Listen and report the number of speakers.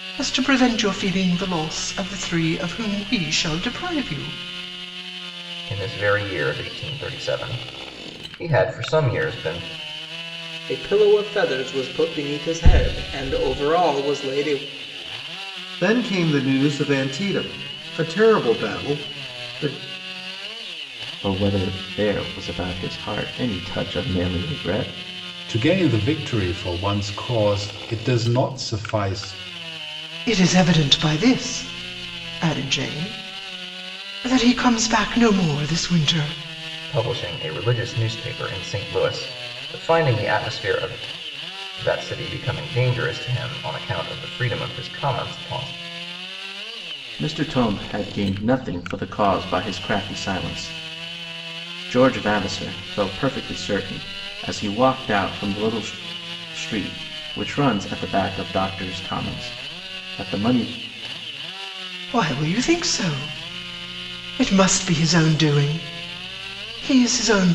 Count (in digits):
6